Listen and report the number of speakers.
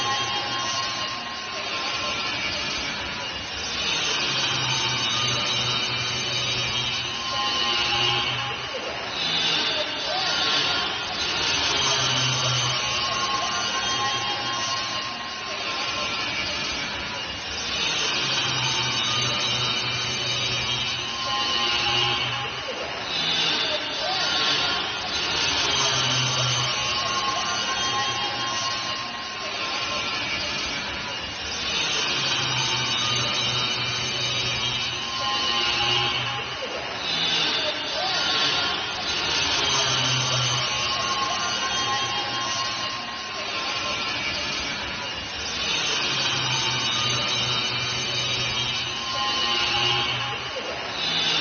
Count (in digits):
0